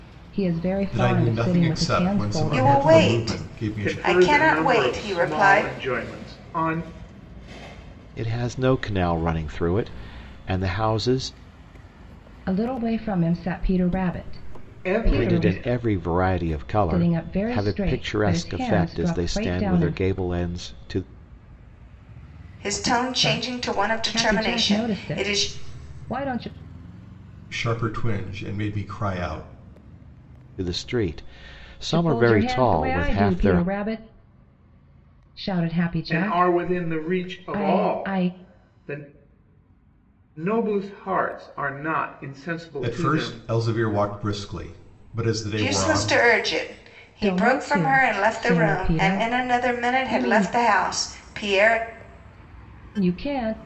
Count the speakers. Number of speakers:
five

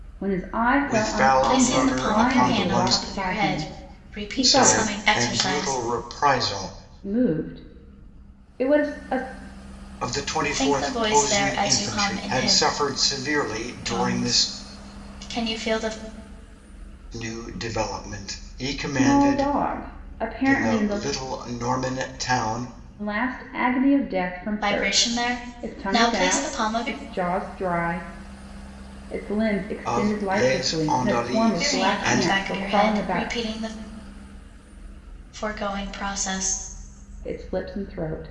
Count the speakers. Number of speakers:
three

